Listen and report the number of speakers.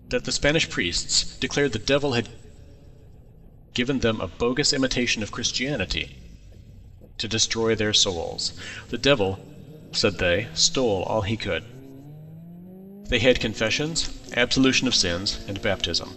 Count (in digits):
1